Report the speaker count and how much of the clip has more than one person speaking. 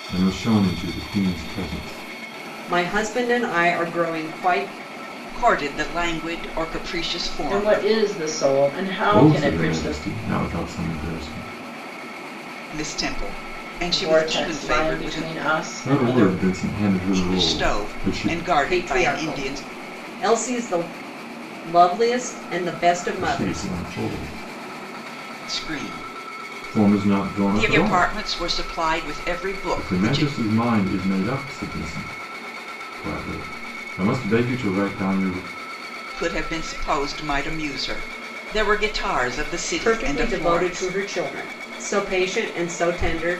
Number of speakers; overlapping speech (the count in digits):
4, about 23%